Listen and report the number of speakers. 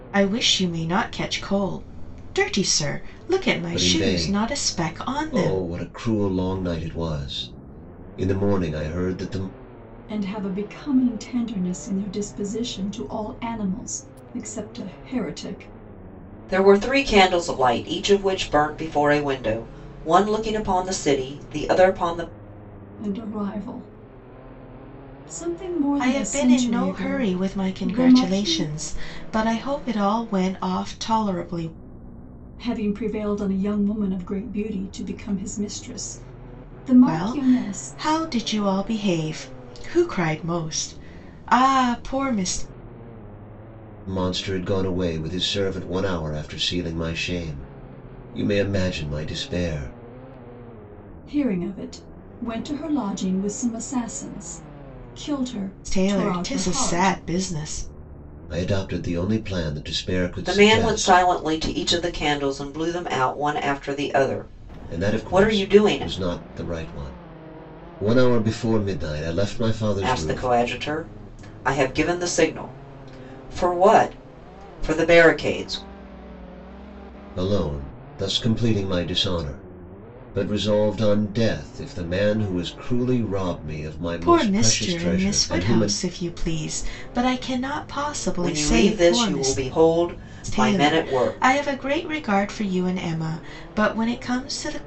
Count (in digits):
4